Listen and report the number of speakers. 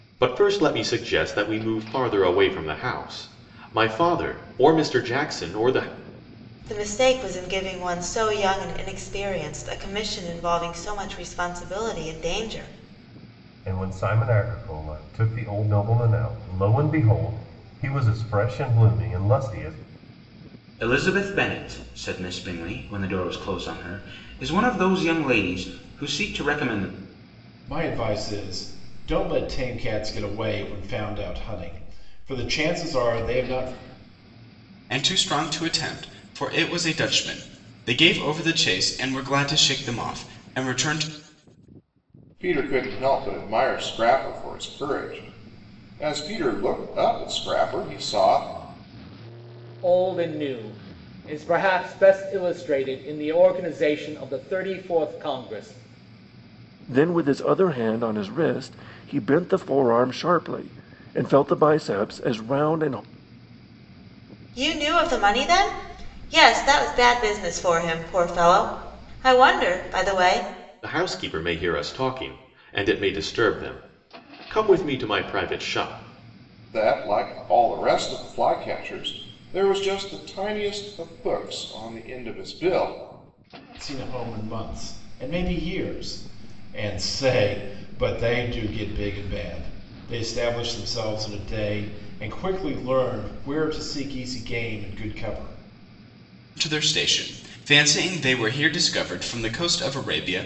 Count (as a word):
nine